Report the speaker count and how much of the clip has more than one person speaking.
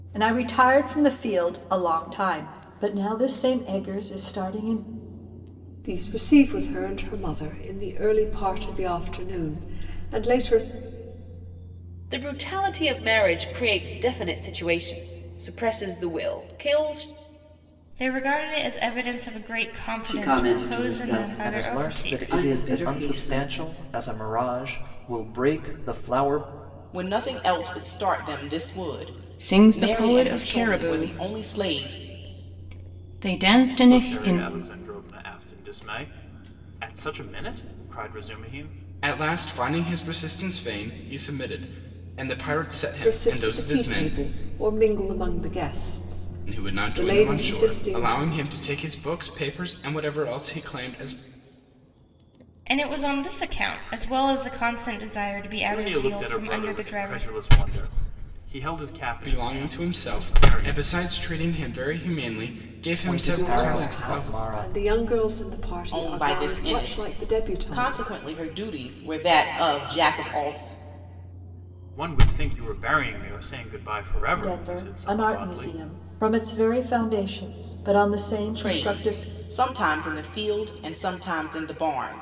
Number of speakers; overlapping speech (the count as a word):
ten, about 23%